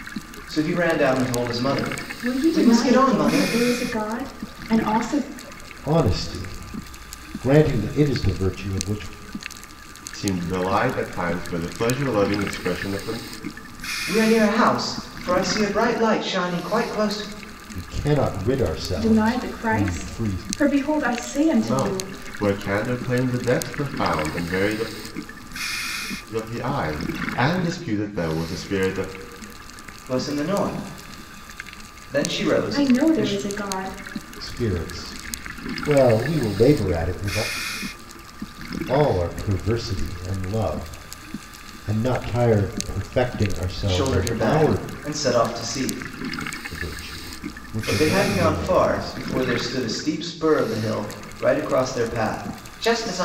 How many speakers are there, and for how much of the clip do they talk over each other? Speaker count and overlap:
four, about 12%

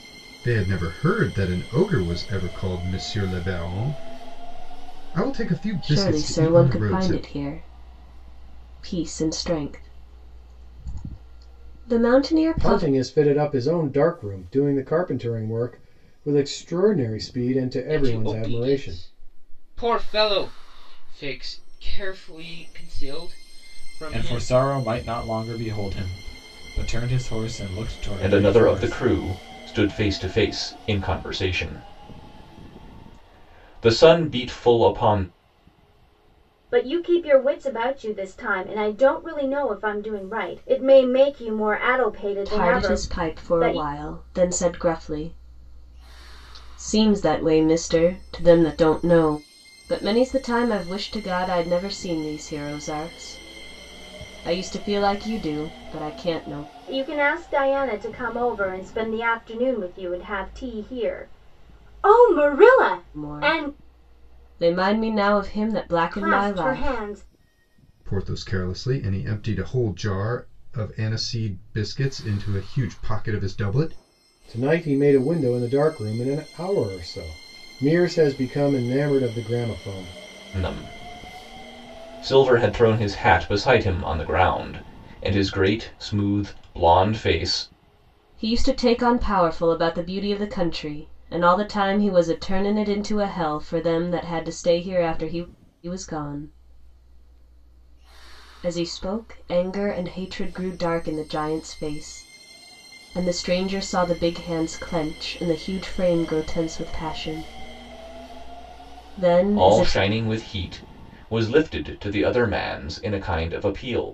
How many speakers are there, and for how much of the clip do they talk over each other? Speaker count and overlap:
seven, about 7%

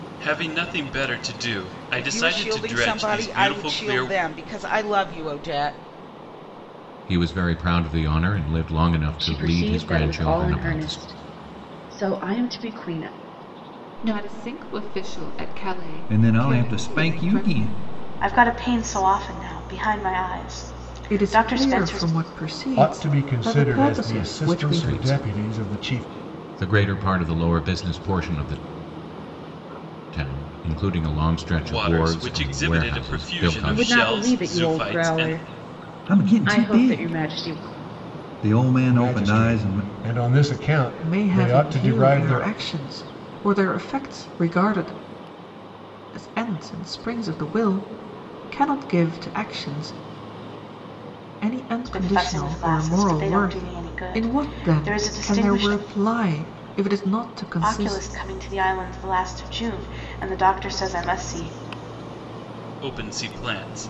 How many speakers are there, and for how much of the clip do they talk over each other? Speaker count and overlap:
nine, about 34%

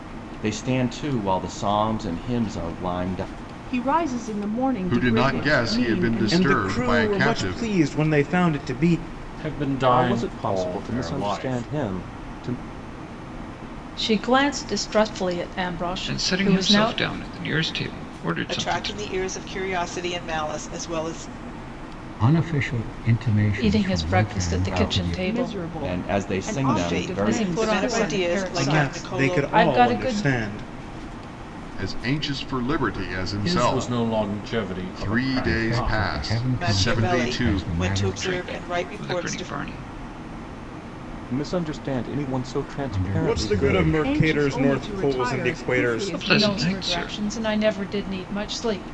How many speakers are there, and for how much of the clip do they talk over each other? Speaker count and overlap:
ten, about 46%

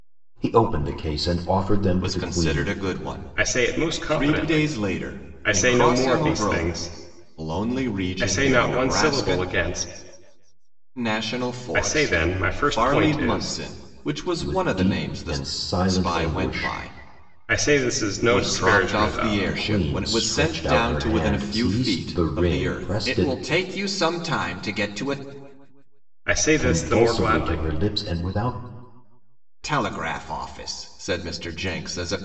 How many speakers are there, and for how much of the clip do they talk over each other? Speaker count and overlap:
three, about 45%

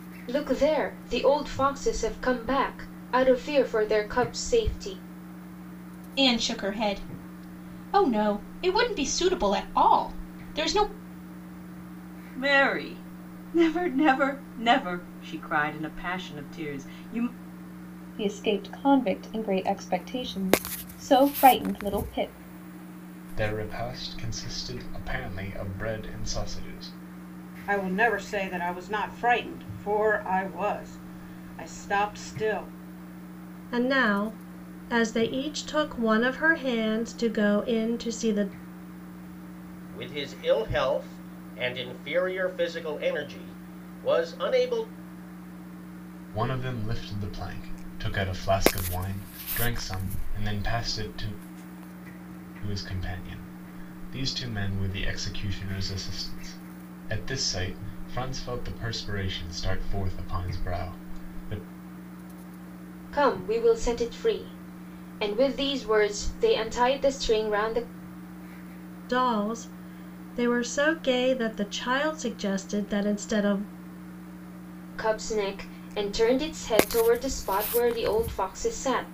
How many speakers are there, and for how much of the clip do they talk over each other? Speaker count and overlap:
eight, no overlap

